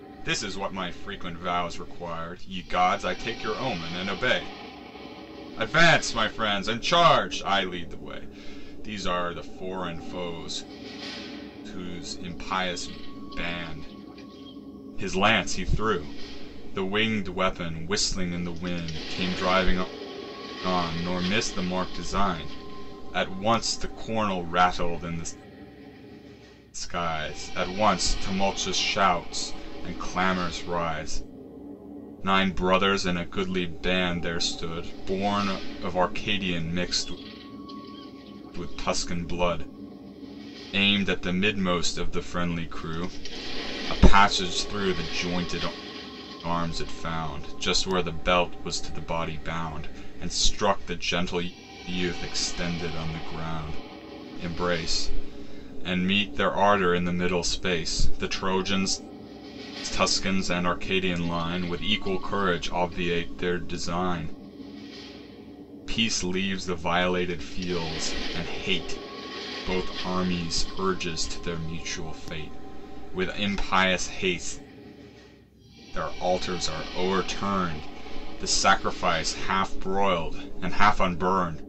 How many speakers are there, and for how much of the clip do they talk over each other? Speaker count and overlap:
one, no overlap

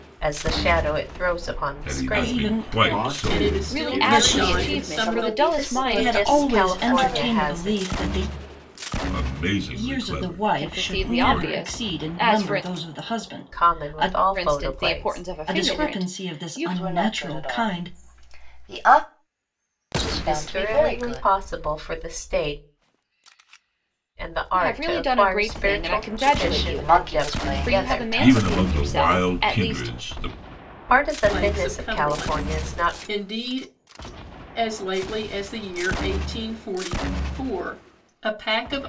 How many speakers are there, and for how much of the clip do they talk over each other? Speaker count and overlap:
seven, about 55%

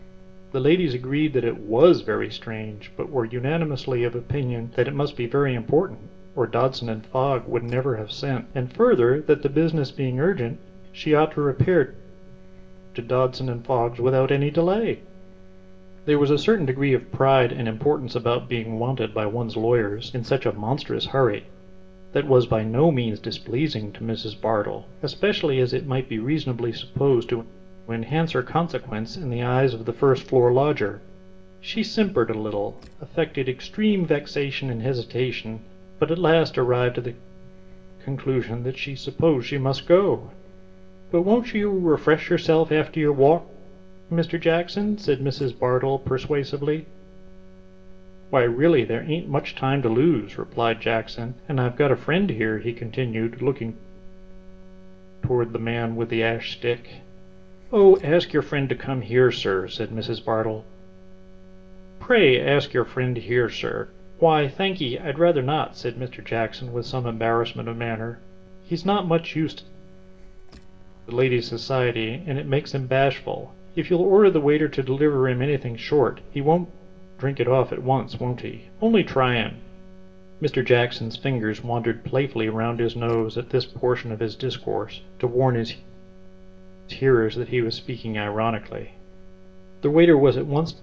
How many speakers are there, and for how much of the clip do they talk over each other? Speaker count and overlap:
one, no overlap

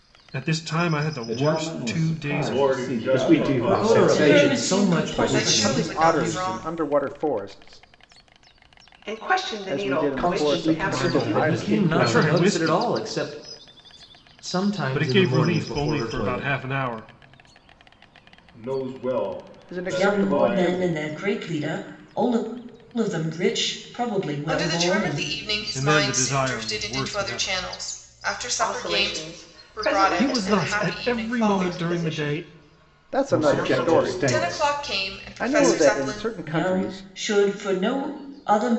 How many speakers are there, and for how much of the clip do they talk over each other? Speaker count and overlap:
nine, about 56%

